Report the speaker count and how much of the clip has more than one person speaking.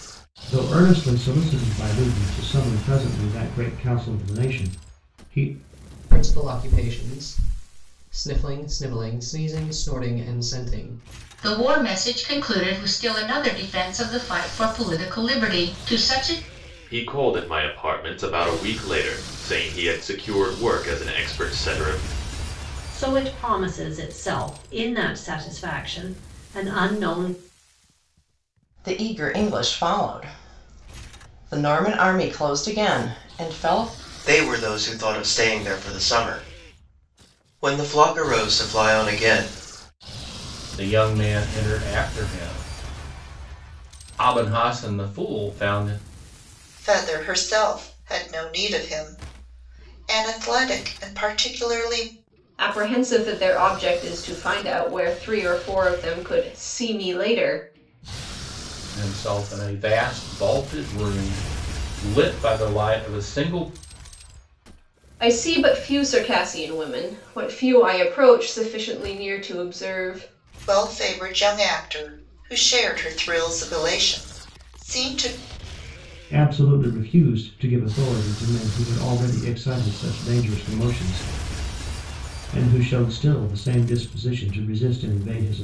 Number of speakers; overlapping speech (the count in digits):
10, no overlap